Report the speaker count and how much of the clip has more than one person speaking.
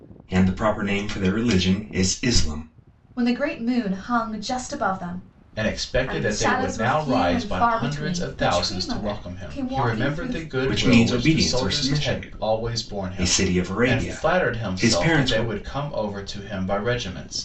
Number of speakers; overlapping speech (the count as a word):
three, about 49%